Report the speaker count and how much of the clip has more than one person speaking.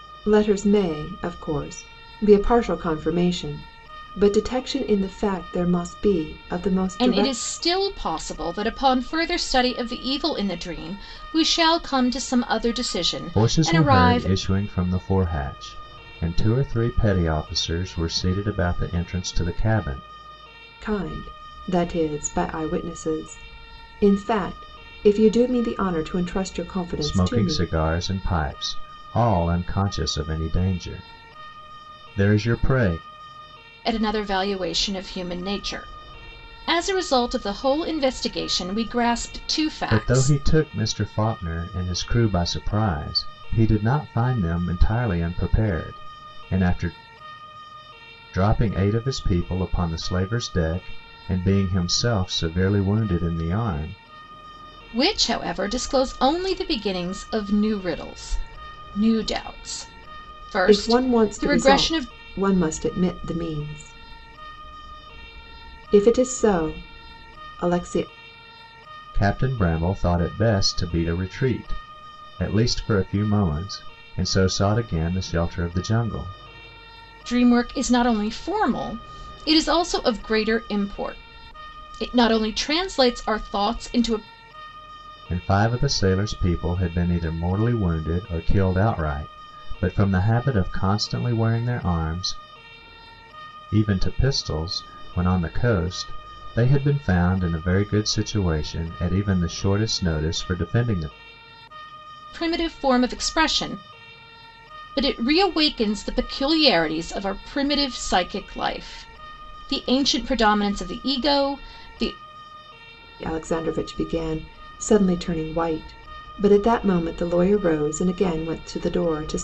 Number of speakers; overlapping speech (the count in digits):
3, about 4%